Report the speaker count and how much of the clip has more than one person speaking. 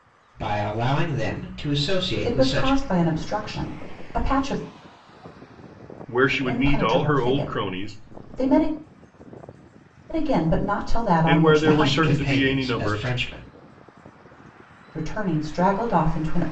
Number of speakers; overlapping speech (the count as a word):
three, about 25%